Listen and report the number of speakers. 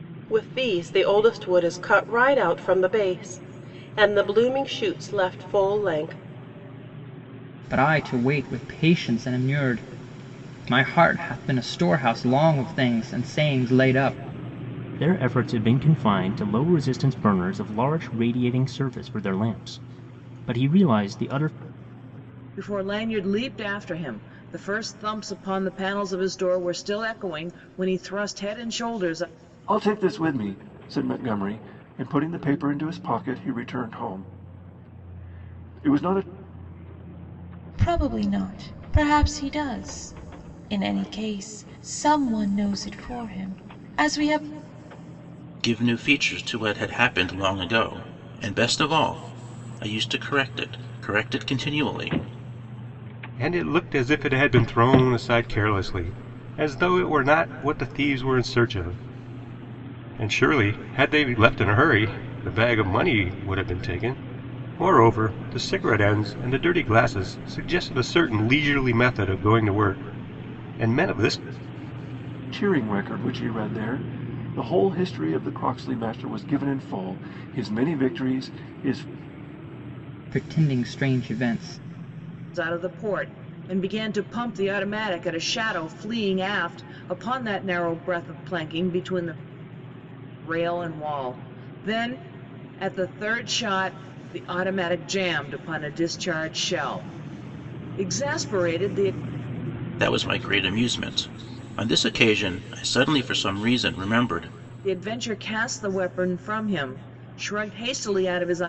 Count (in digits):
8